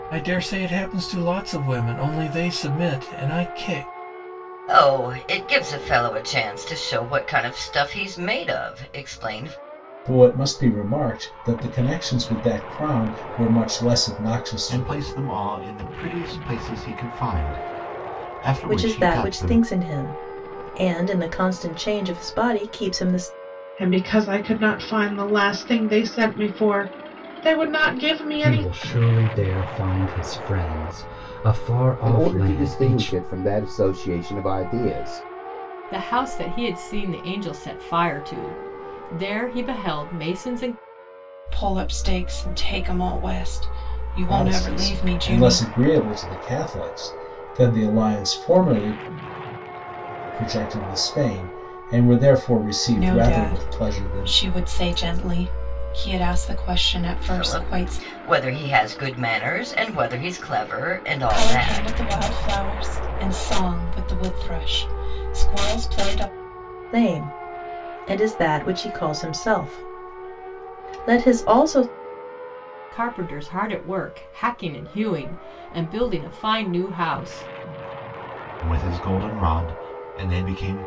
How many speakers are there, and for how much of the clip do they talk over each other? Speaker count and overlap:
10, about 9%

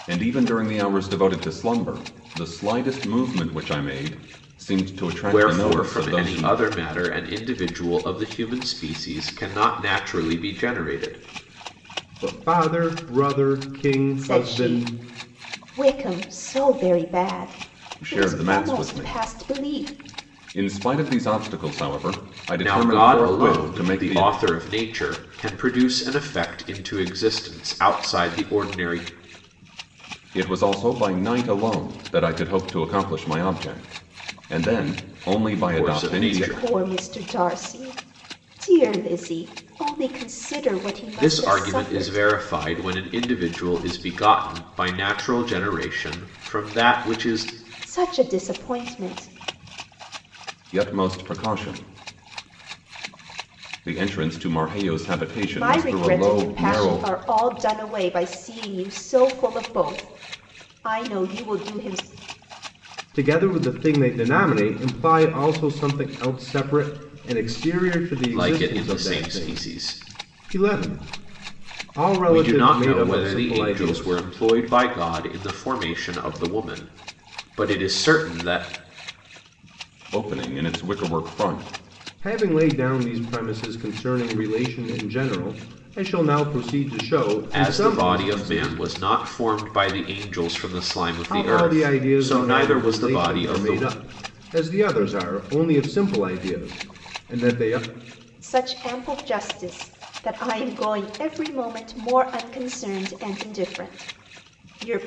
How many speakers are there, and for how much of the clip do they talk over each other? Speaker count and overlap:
4, about 16%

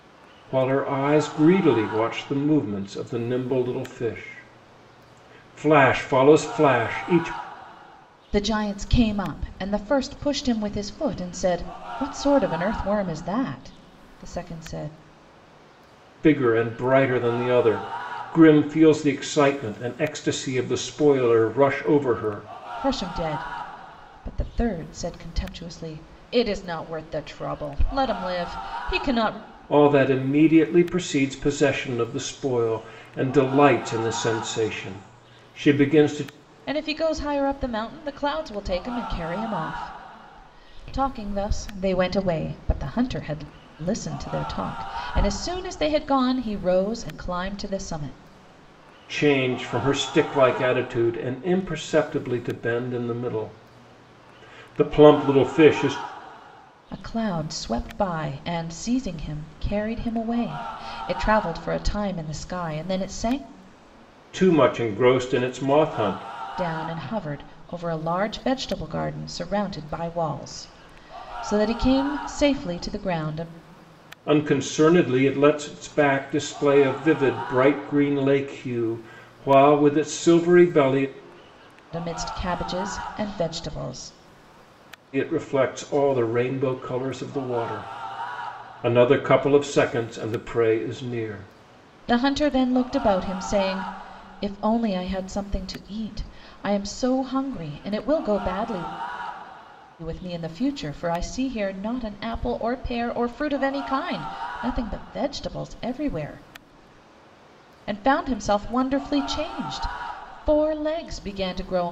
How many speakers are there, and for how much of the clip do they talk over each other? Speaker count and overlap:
2, no overlap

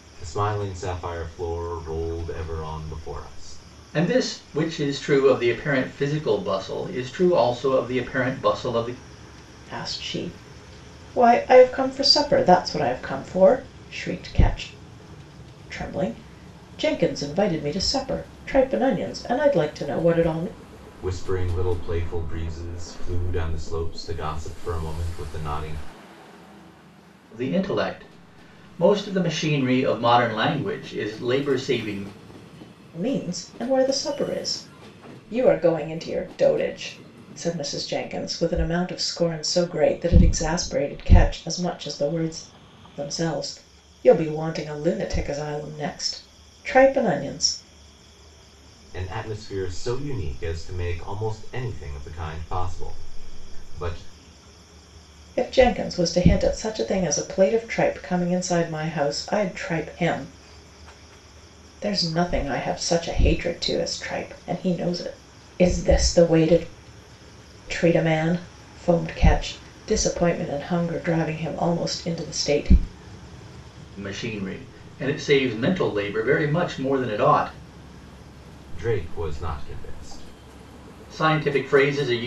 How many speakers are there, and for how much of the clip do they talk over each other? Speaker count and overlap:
3, no overlap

